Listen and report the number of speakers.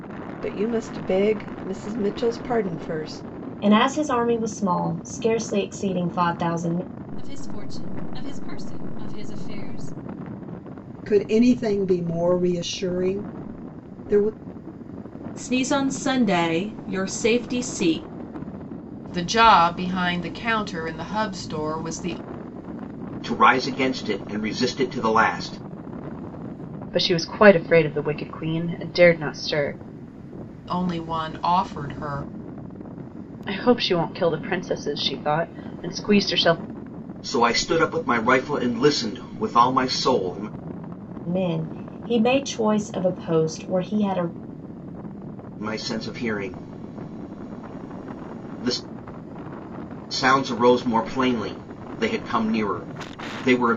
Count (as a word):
eight